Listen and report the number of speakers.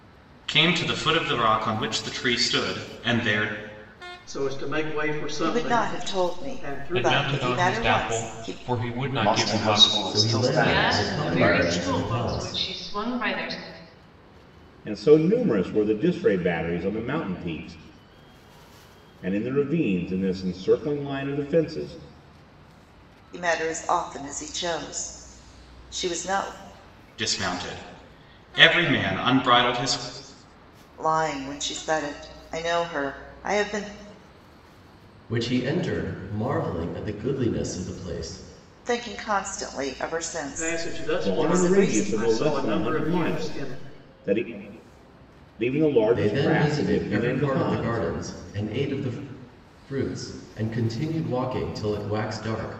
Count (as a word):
eight